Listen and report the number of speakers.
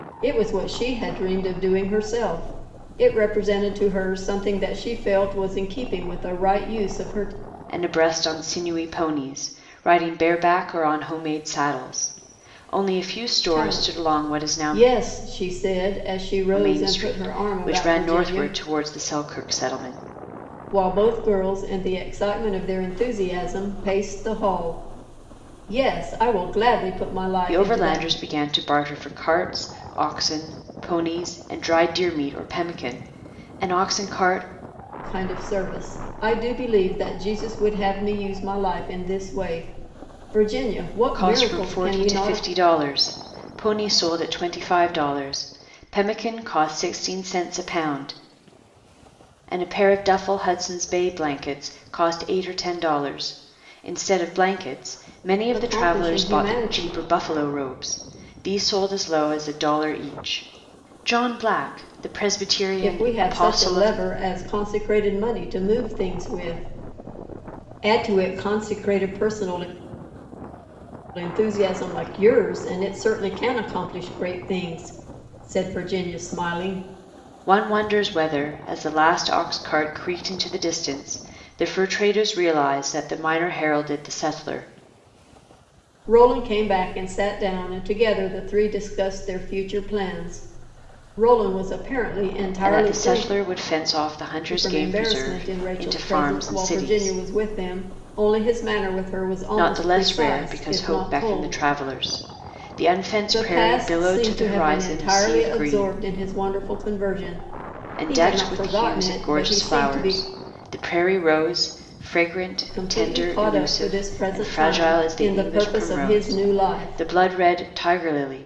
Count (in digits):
2